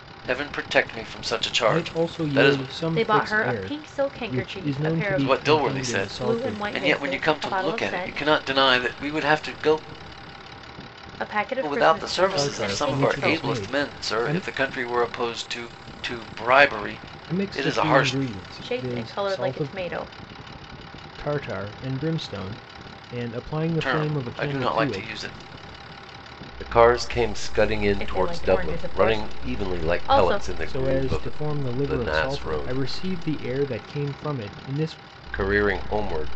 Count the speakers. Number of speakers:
3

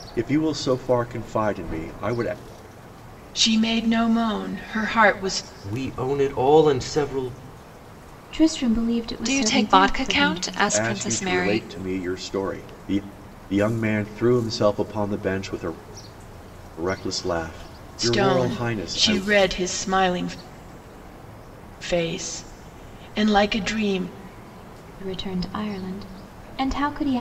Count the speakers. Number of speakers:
5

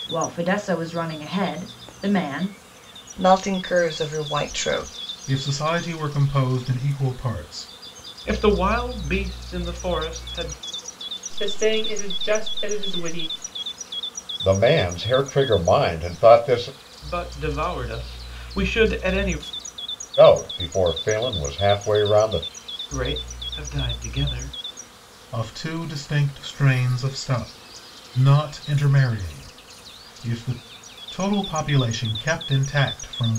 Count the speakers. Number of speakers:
6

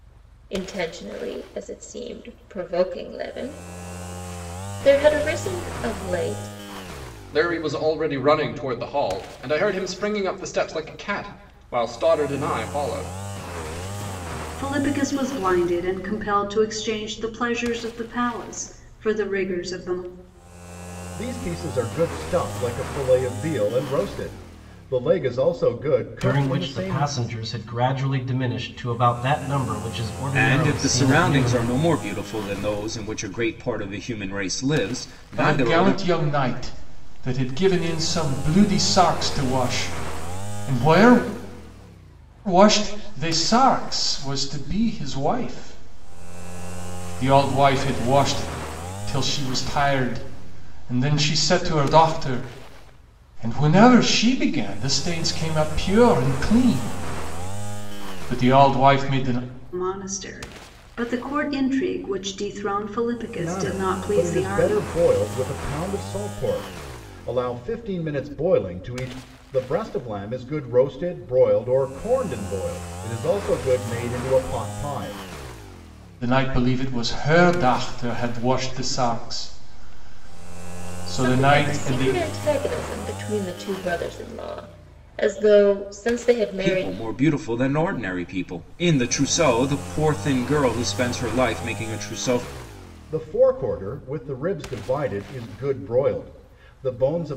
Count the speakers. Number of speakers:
7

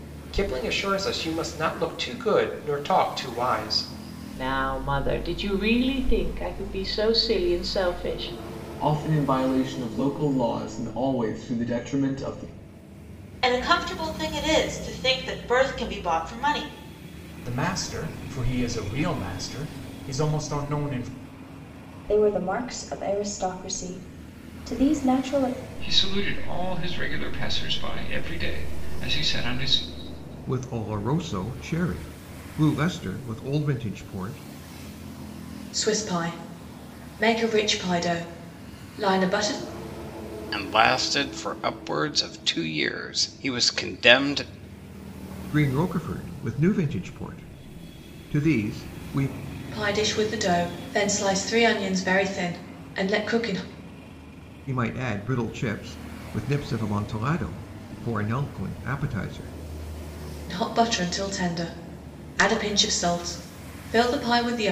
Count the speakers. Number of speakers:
10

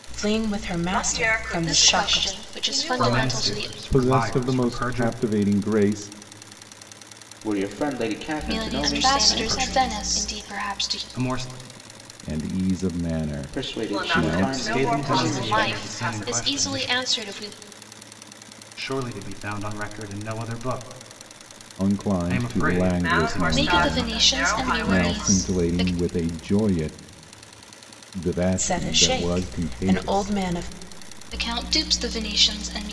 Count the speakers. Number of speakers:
7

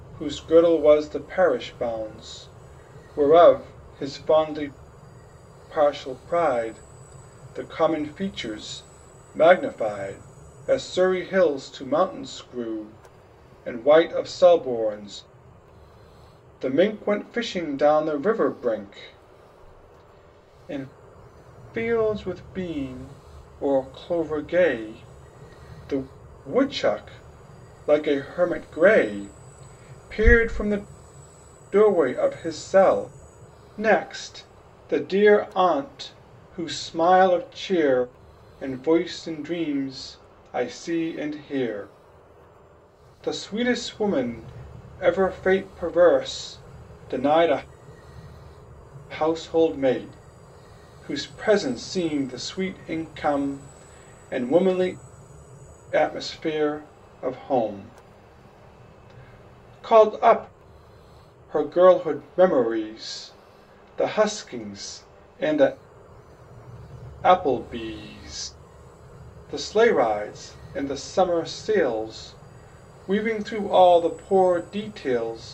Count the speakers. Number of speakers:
1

